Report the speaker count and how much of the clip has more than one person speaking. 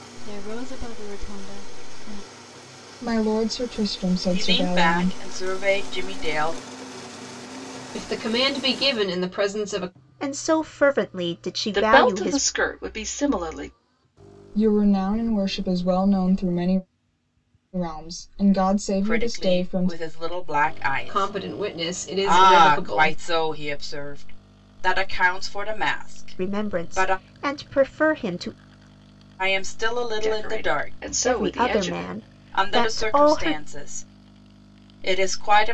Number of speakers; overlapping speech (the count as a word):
six, about 22%